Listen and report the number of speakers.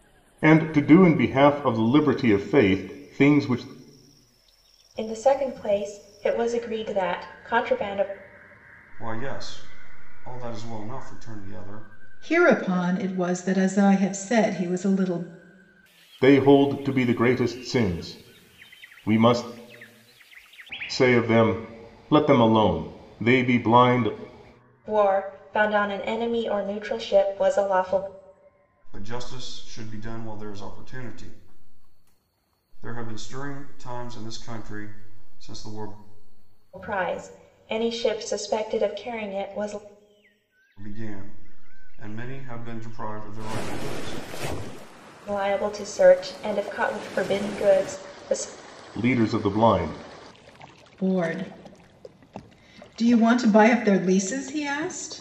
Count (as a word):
four